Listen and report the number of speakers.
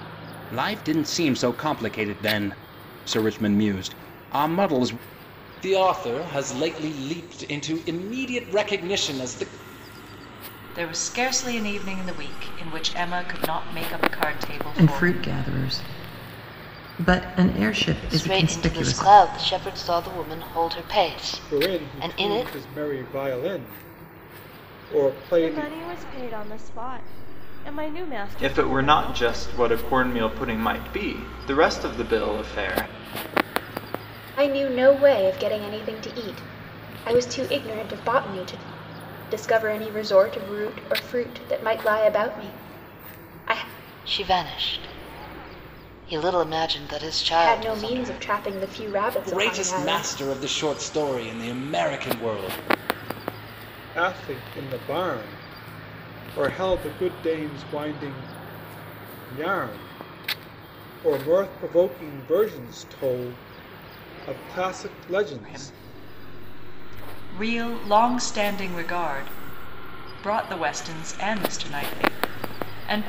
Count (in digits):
9